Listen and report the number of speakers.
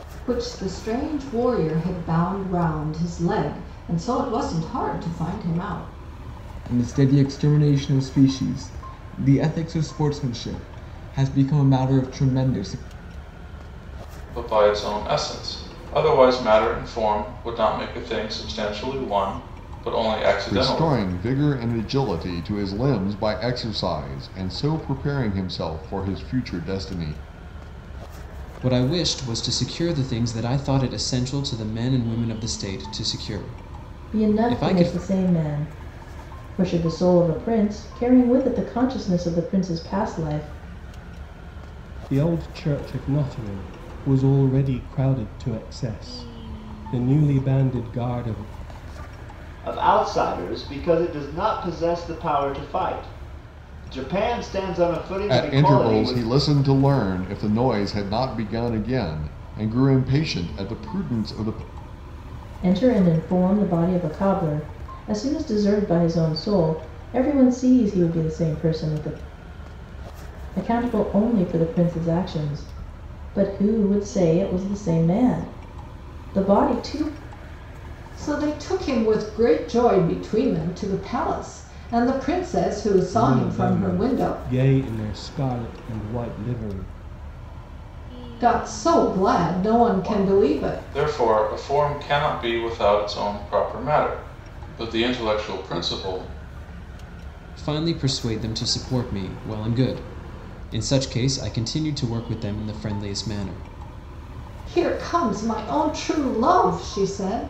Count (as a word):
eight